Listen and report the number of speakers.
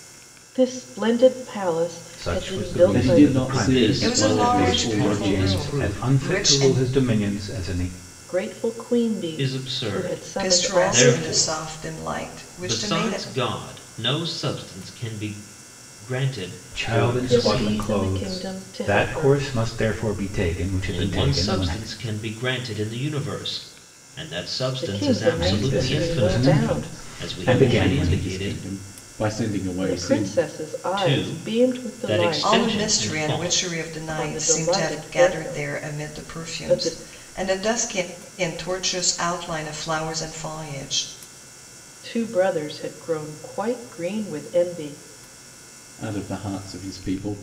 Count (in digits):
5